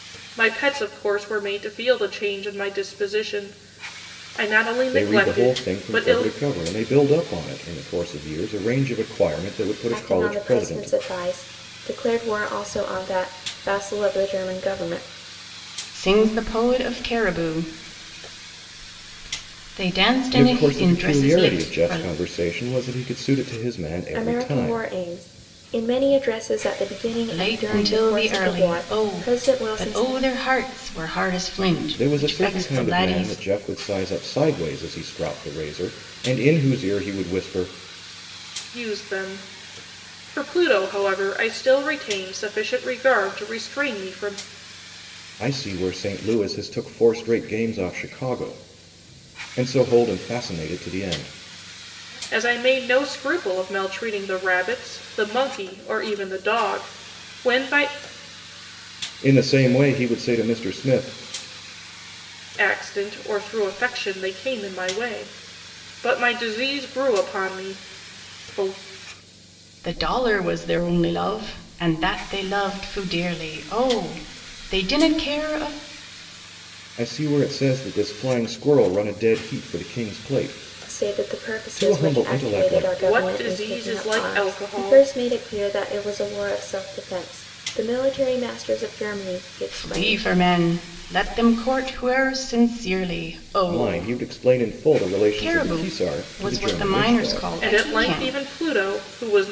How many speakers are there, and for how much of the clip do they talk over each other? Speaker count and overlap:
four, about 18%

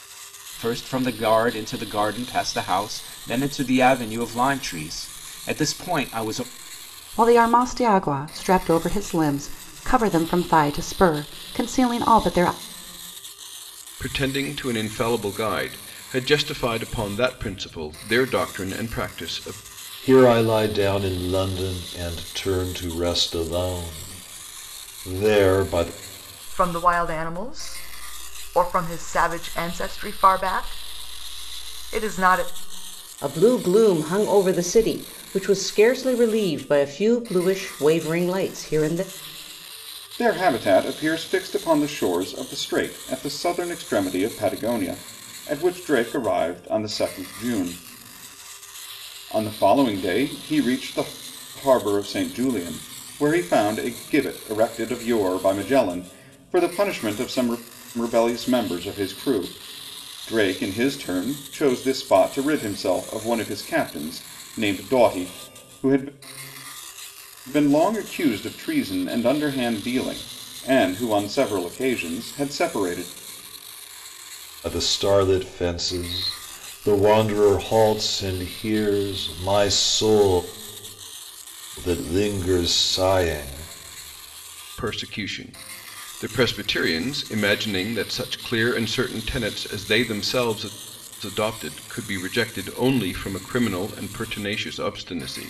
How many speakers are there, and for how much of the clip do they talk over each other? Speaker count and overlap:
seven, no overlap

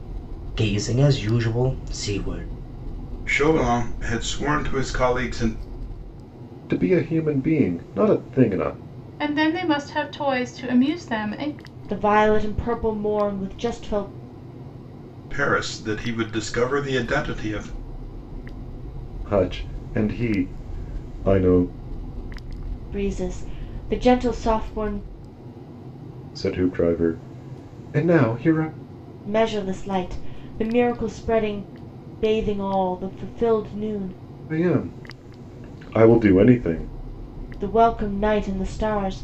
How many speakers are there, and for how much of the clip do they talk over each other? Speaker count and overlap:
five, no overlap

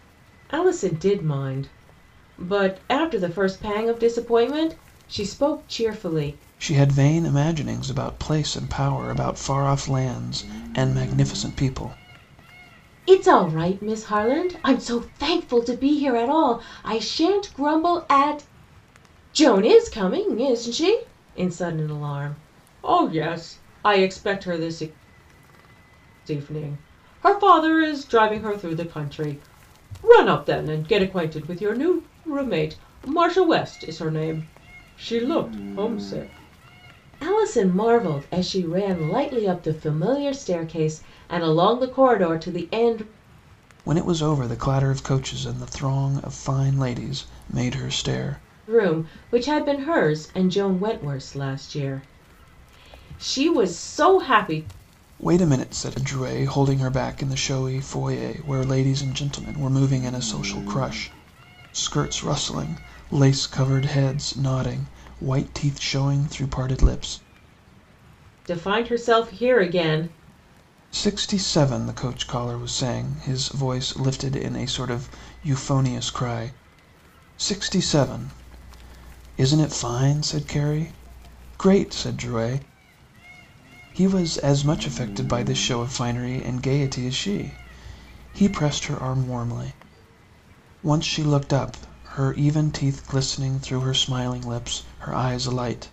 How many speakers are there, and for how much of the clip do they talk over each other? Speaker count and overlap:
two, no overlap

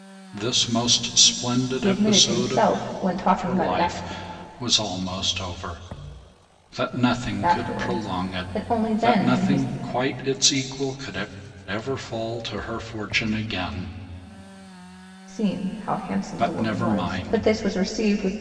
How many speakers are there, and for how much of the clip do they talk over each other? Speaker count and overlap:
two, about 25%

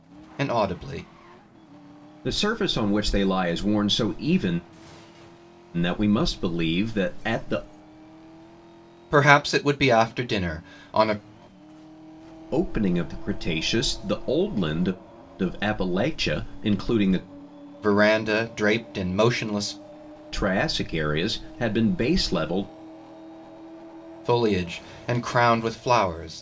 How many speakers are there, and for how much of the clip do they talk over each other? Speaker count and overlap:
two, no overlap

